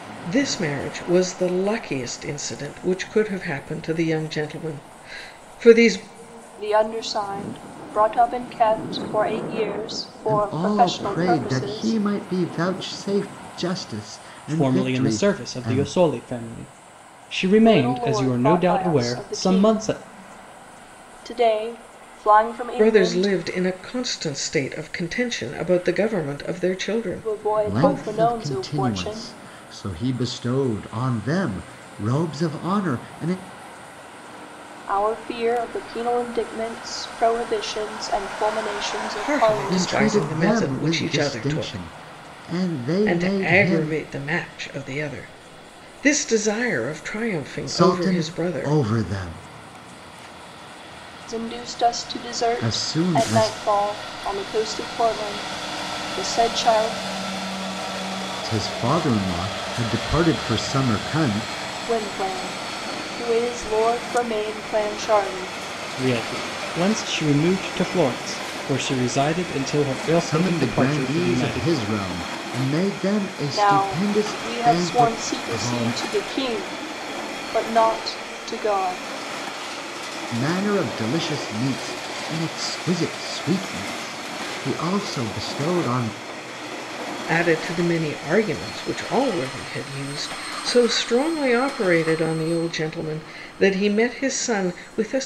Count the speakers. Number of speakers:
four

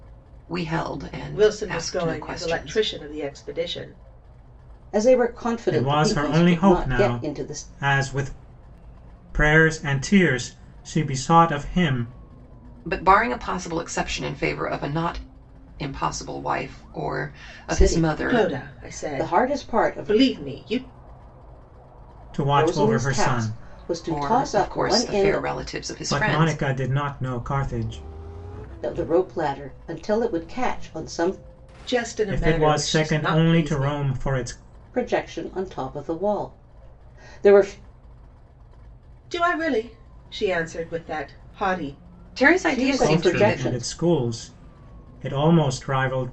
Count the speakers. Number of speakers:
four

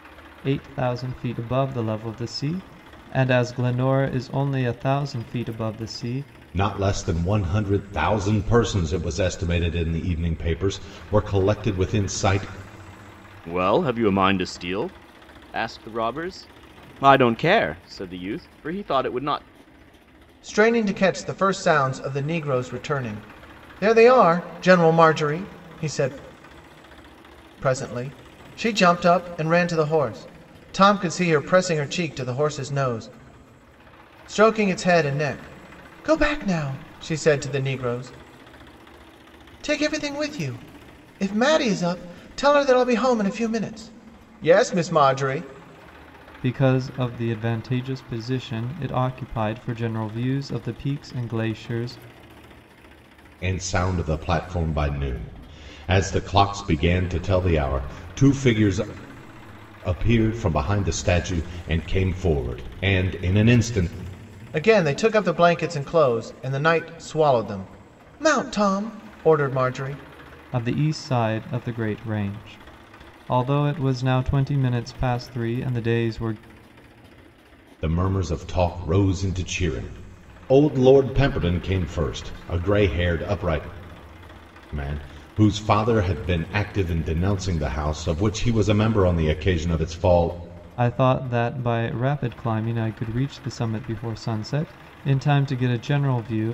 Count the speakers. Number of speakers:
four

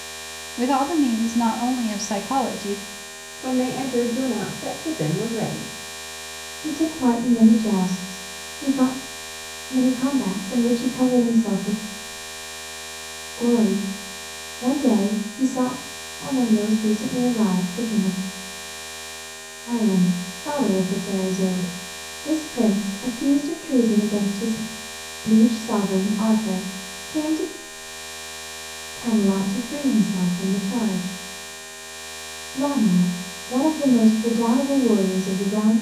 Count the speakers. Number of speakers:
three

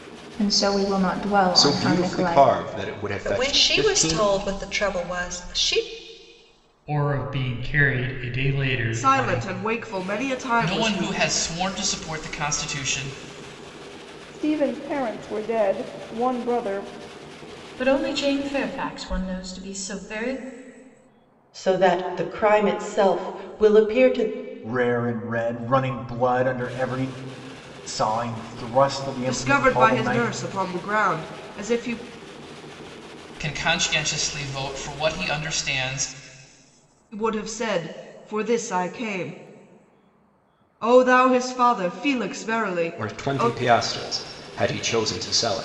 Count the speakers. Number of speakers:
ten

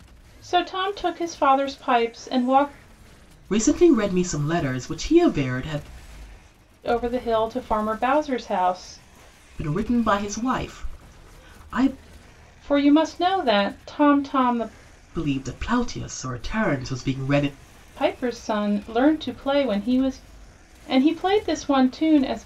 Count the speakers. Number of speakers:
two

